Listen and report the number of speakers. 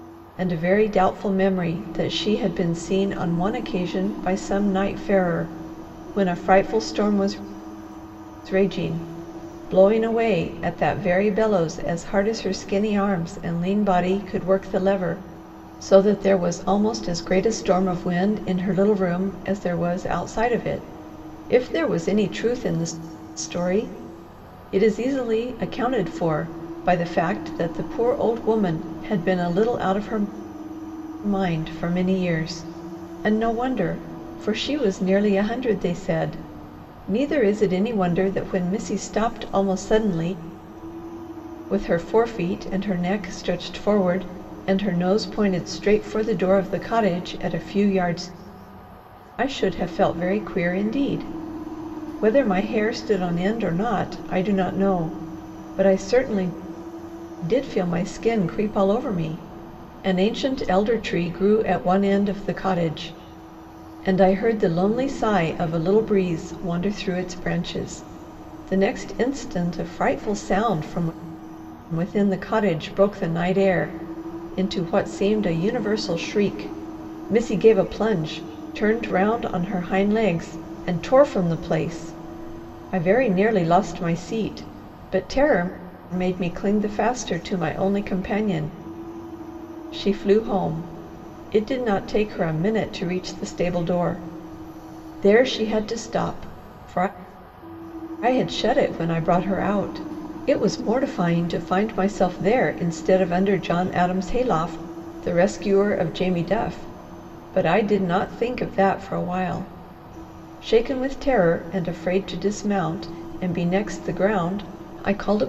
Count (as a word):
one